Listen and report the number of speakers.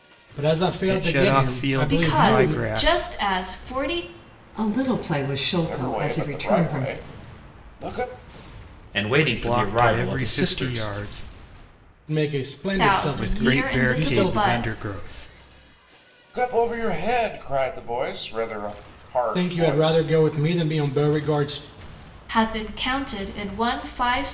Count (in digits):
6